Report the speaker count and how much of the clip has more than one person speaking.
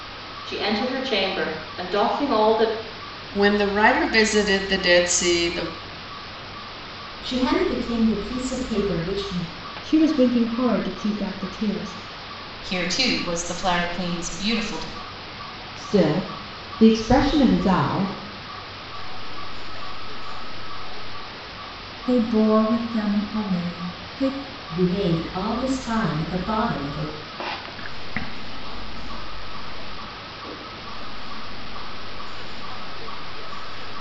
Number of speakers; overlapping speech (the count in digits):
8, no overlap